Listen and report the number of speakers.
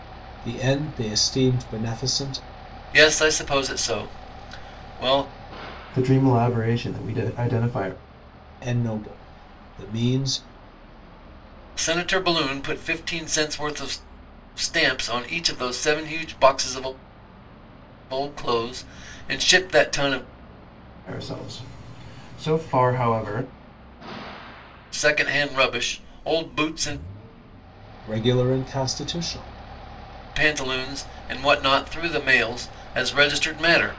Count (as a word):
three